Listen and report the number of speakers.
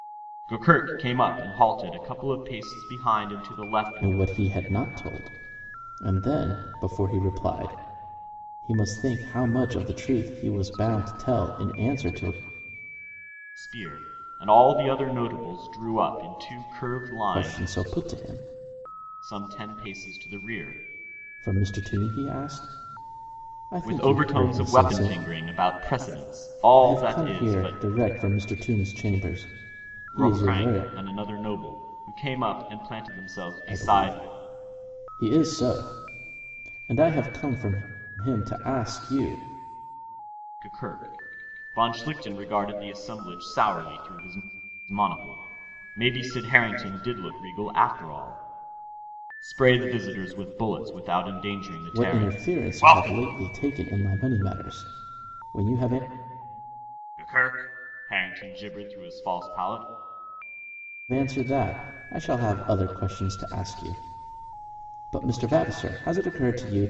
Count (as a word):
two